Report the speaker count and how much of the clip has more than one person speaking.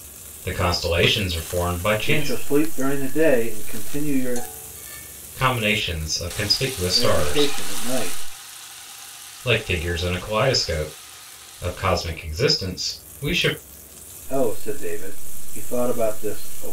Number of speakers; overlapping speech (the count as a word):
two, about 6%